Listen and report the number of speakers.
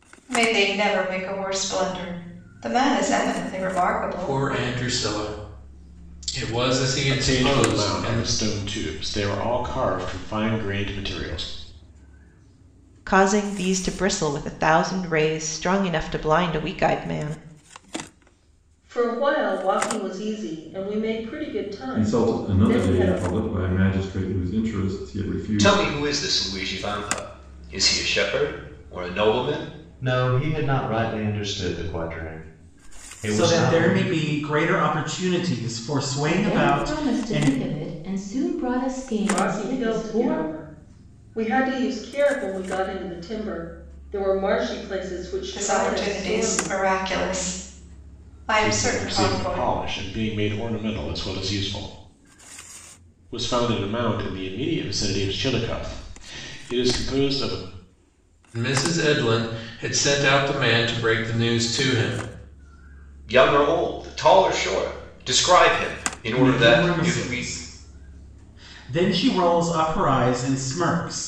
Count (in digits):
10